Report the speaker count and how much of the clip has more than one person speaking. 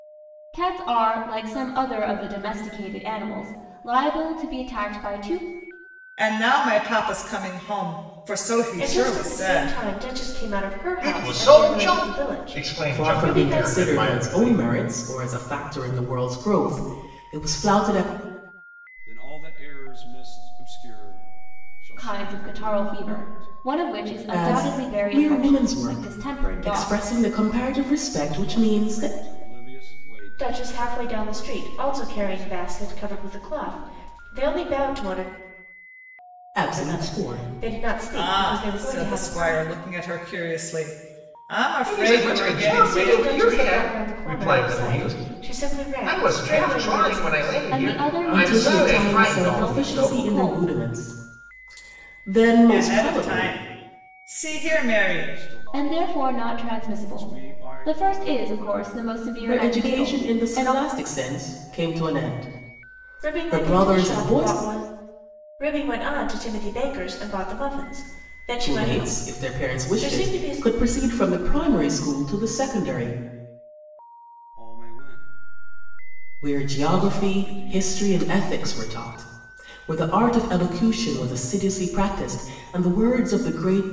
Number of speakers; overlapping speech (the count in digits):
6, about 42%